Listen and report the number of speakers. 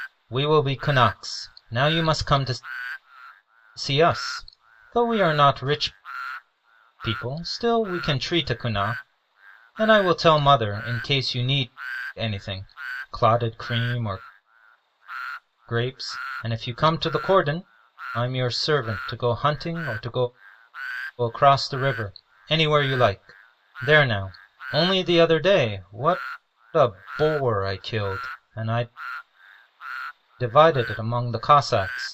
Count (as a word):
one